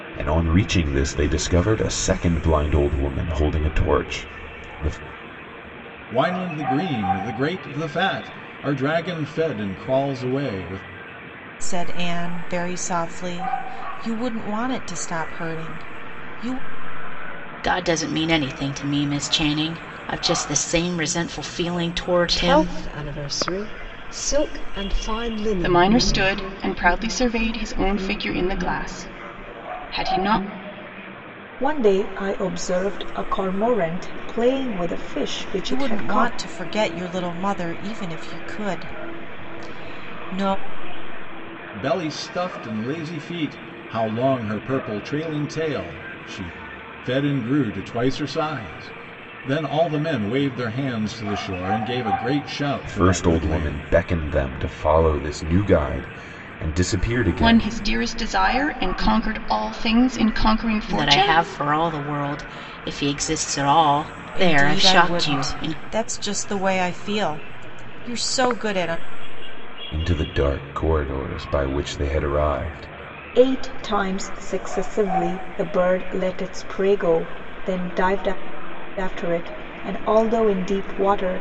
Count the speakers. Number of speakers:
seven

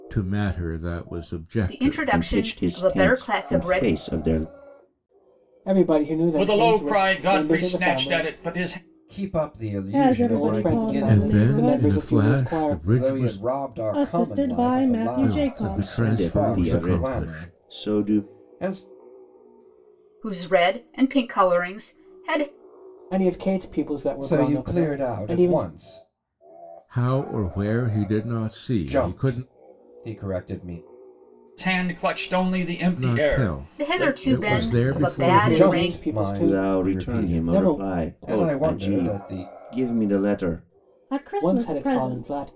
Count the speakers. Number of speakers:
seven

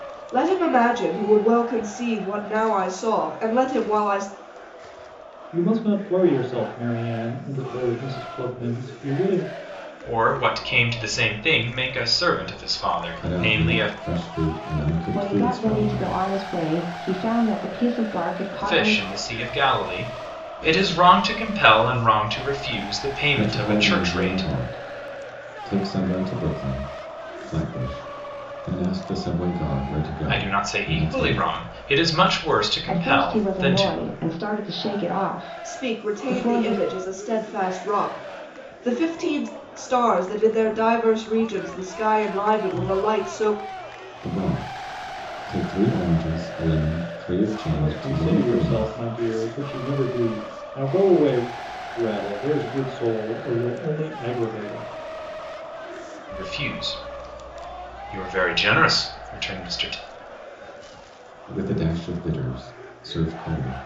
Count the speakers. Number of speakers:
five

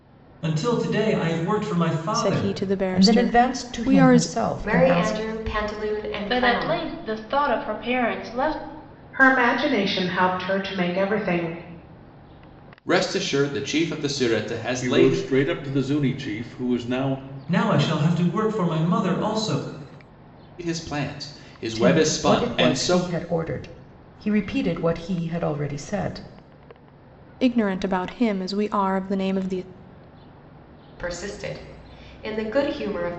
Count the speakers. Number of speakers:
eight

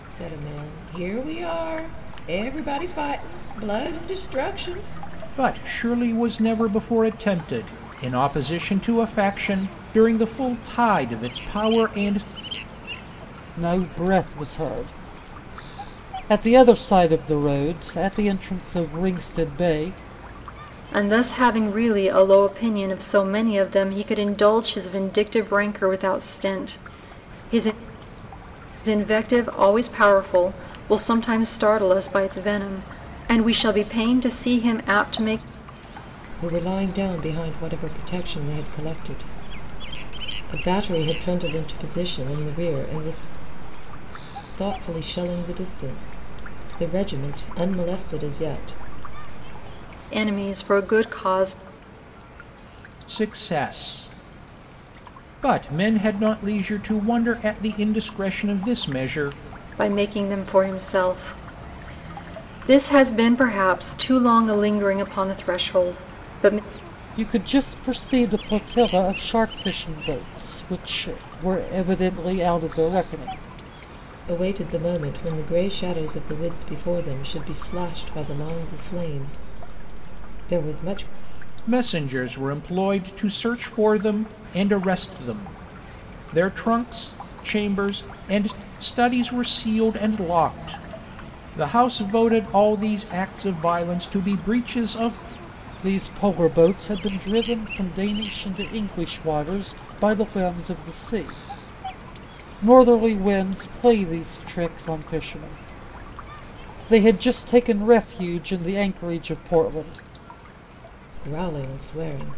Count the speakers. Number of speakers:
four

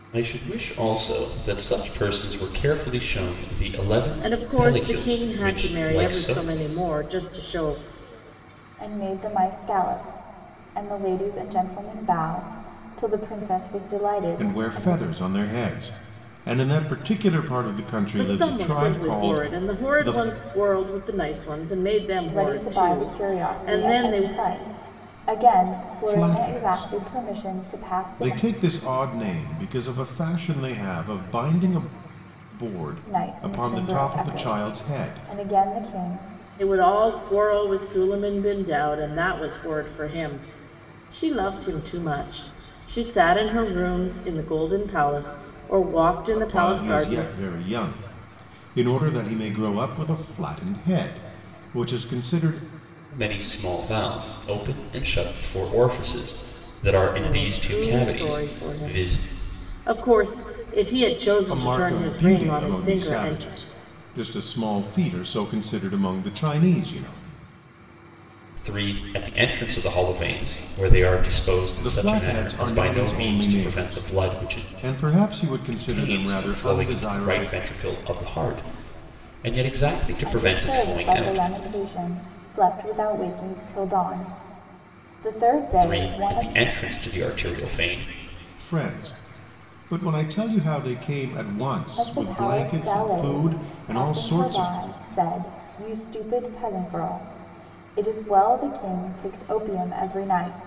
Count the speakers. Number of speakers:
four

